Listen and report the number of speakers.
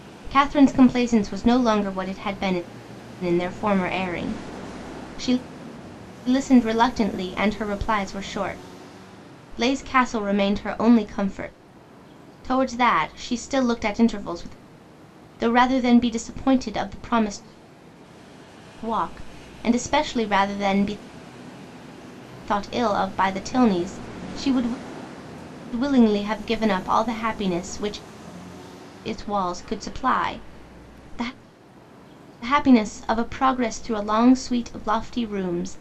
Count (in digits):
1